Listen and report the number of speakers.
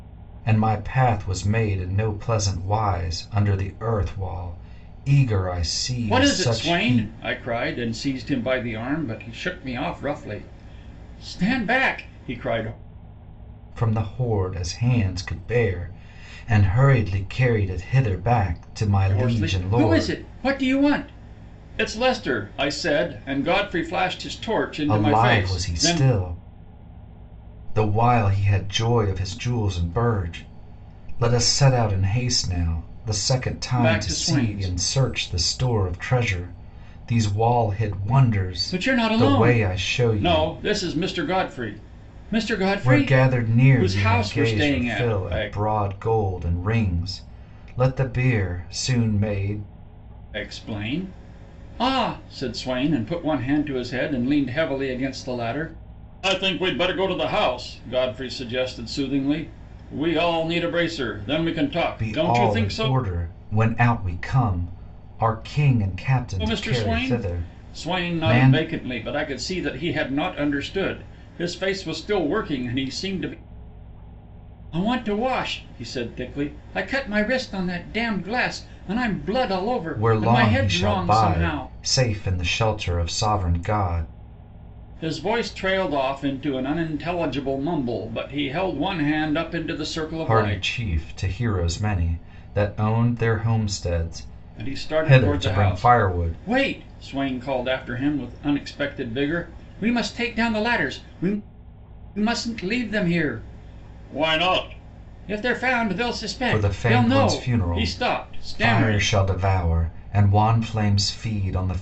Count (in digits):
2